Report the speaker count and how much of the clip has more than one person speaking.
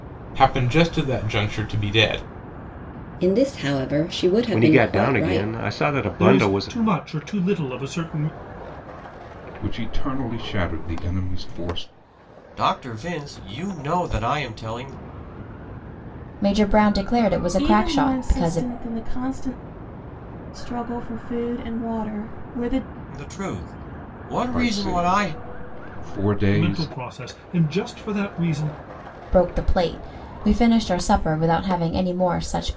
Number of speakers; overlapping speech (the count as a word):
eight, about 13%